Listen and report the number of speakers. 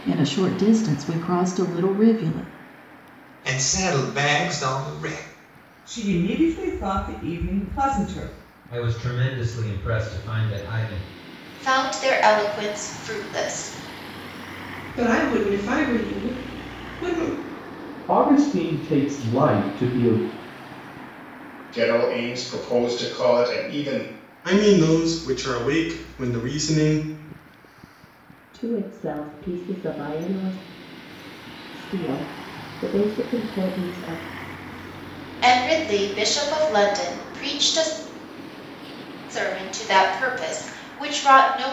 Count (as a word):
ten